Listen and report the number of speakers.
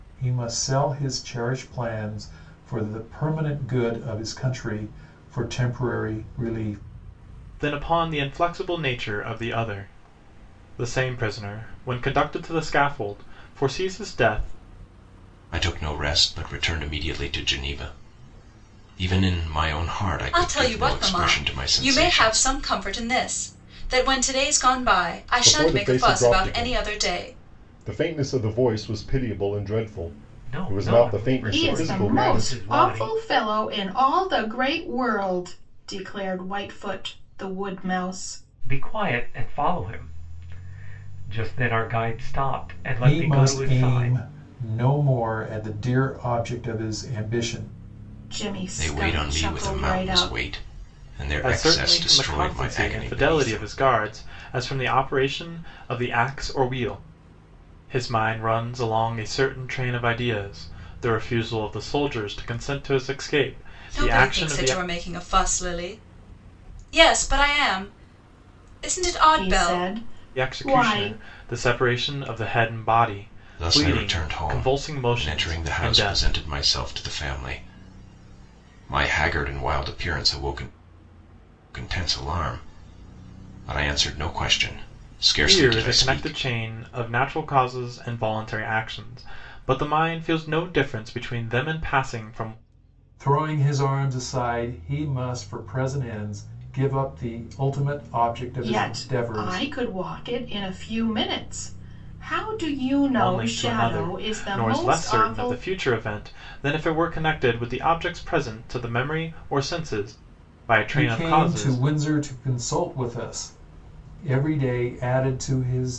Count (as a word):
seven